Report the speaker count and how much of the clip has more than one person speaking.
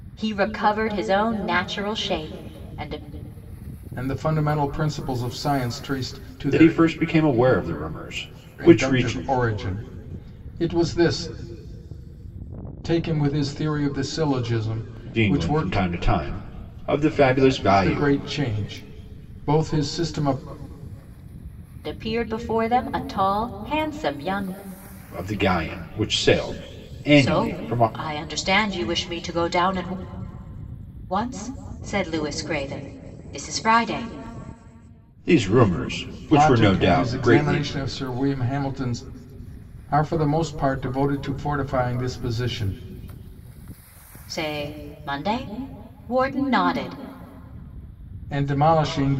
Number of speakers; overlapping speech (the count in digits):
3, about 9%